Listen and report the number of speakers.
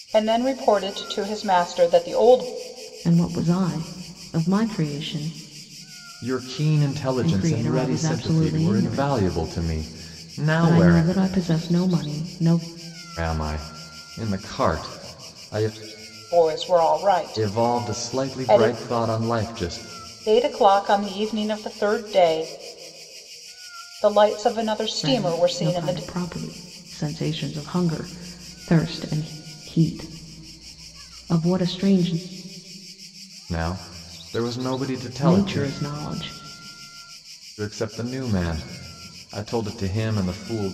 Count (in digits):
3